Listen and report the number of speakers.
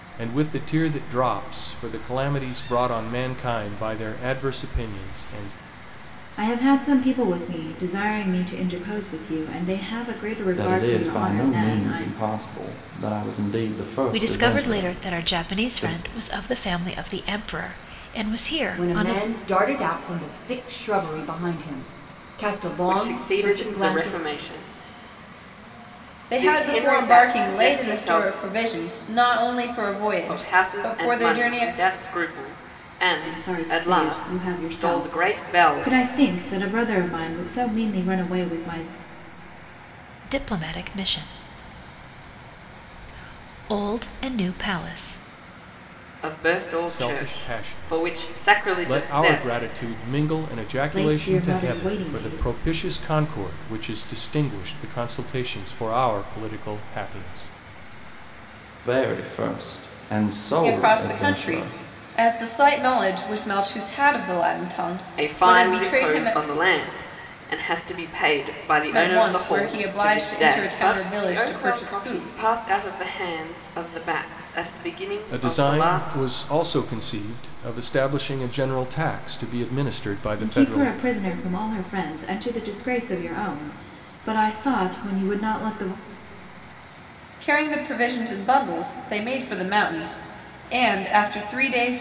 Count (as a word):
seven